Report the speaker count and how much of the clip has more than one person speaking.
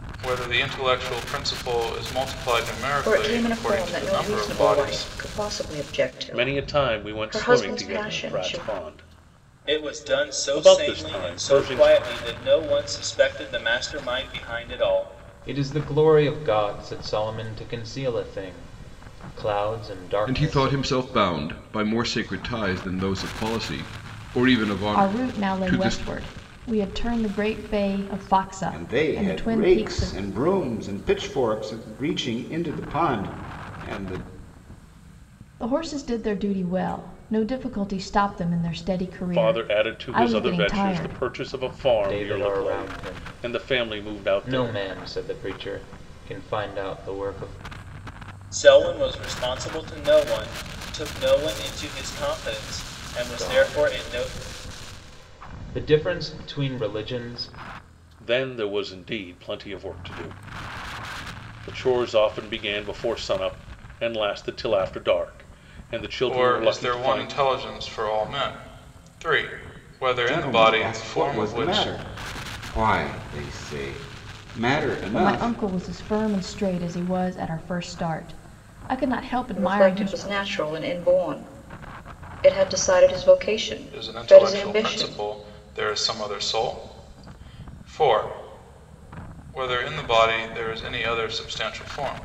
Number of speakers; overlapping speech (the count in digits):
8, about 23%